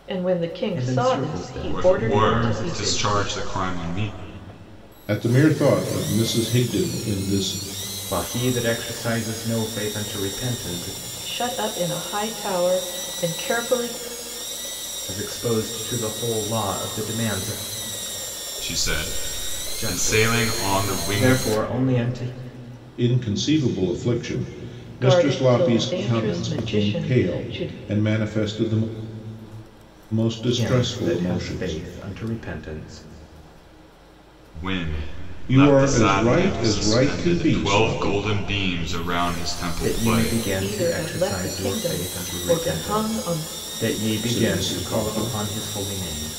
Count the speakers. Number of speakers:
four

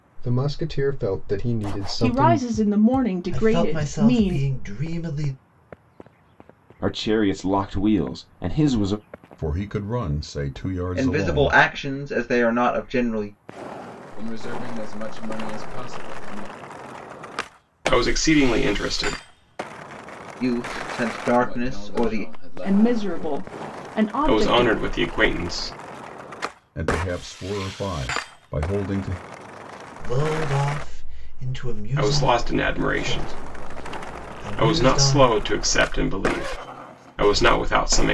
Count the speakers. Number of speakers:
eight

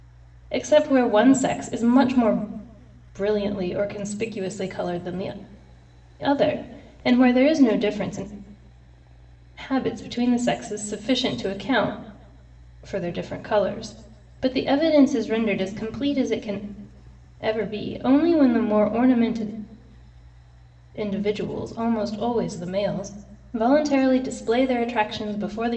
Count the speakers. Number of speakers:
one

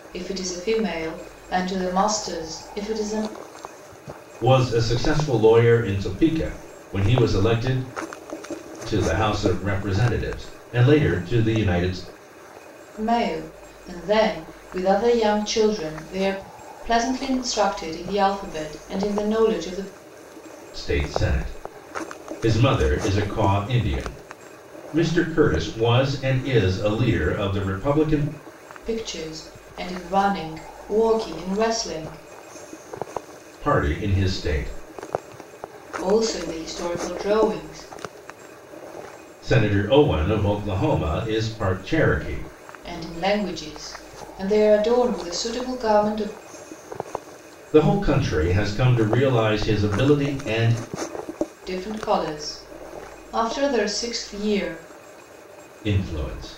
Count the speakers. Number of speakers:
two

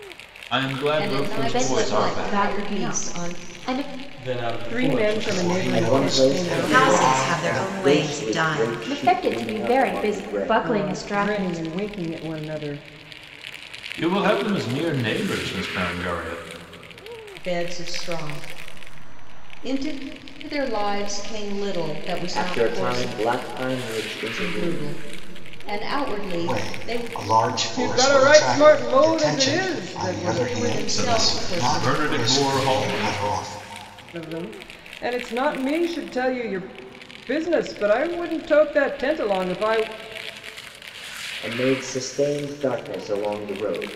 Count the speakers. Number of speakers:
eight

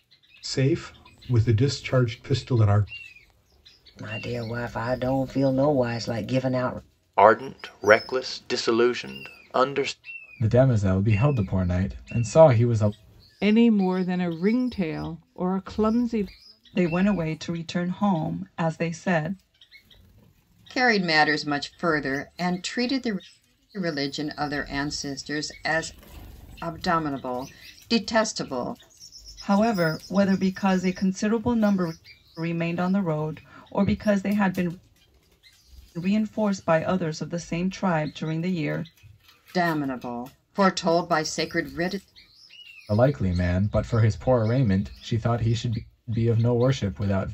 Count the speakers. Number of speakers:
seven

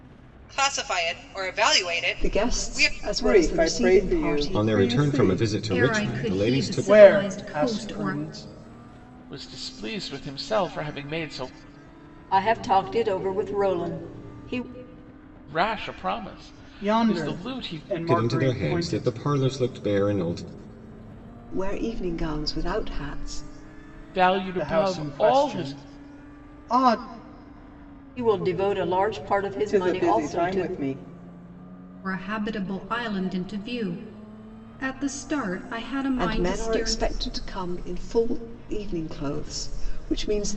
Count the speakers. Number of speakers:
eight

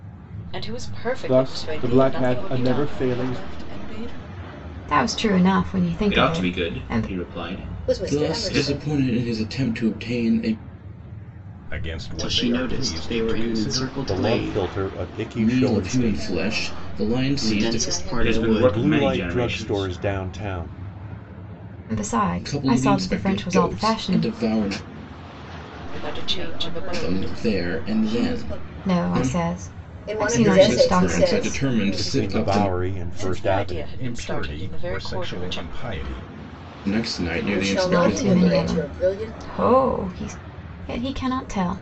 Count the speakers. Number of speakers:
ten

